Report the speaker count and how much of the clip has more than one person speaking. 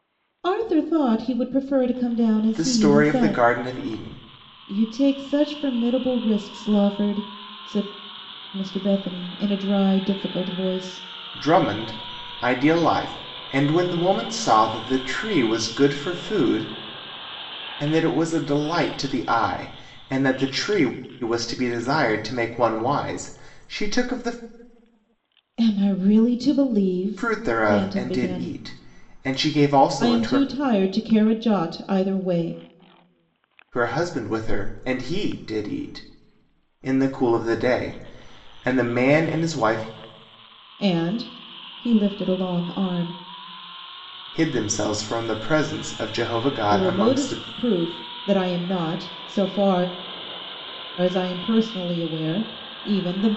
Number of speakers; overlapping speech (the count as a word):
two, about 7%